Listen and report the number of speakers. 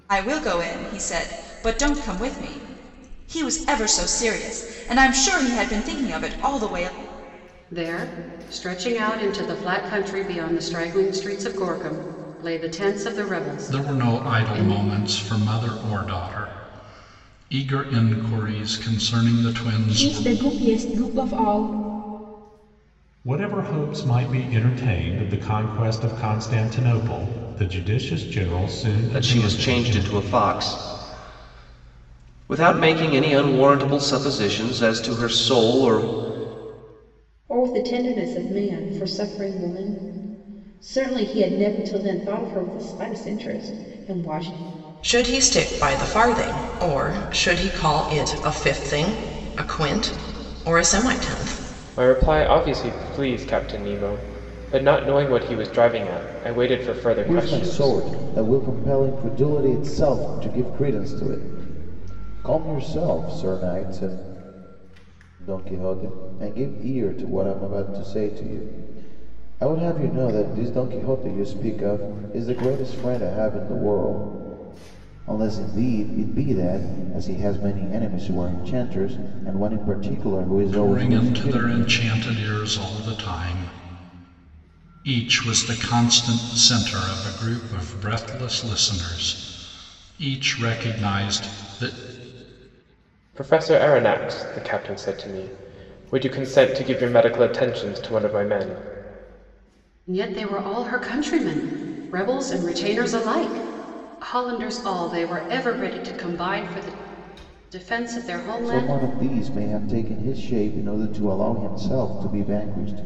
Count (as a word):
ten